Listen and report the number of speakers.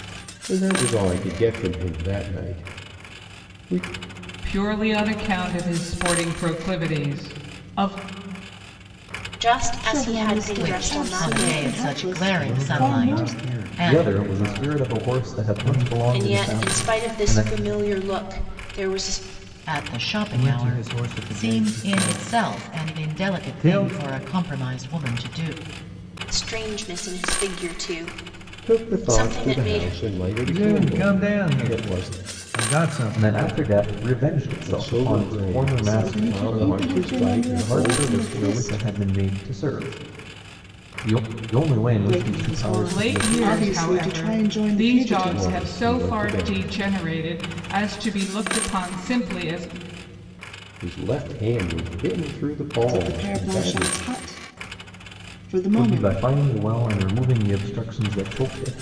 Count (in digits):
7